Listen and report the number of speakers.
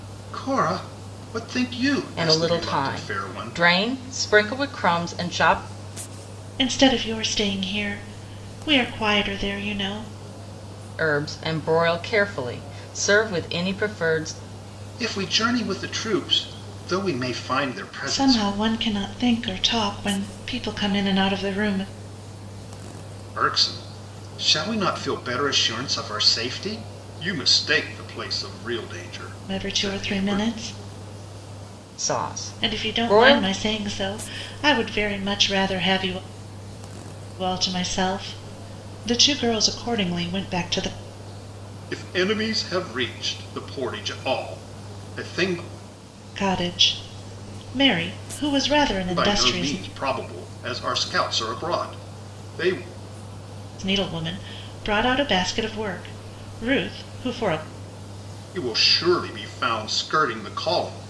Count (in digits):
3